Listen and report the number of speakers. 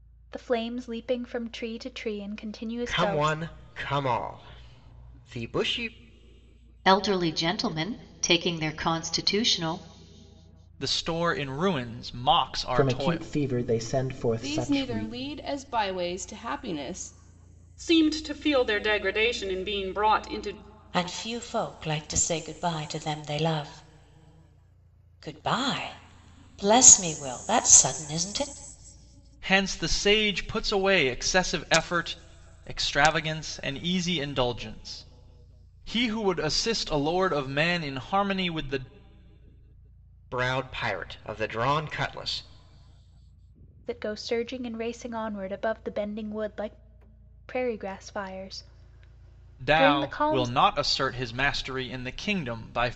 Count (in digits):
8